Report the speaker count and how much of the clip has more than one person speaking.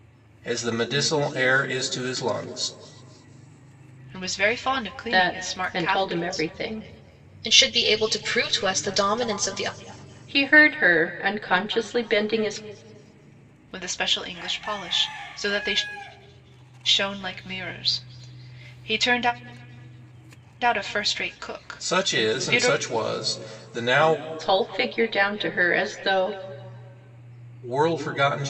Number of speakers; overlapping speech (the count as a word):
four, about 9%